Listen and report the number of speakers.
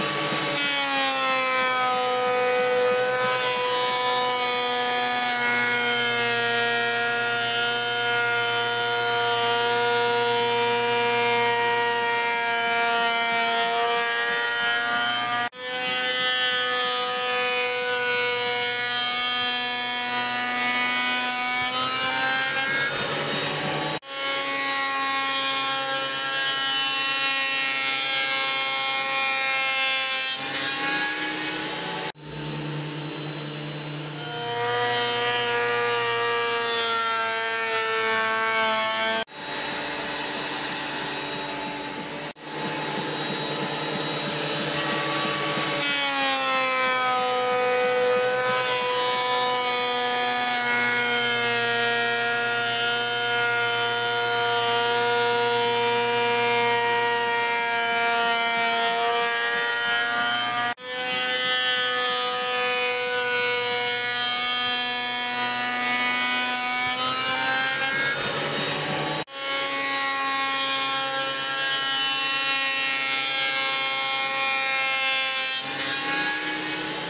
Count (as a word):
zero